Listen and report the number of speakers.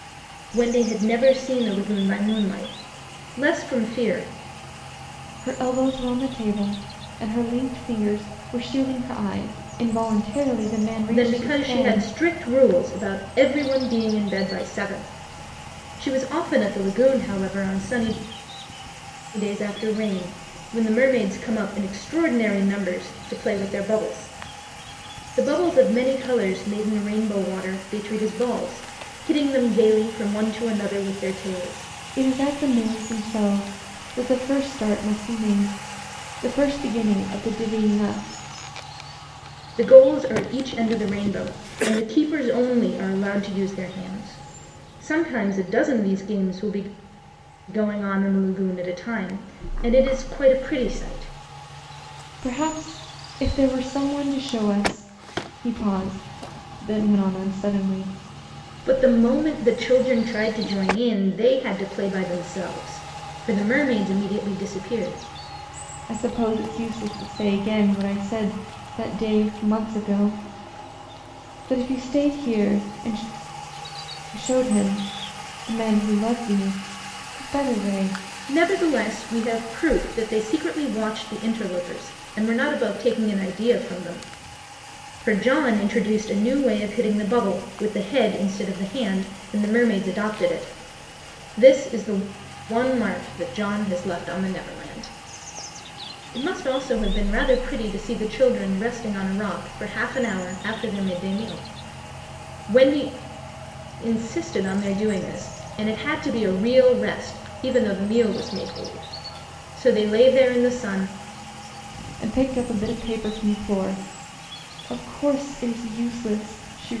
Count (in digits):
2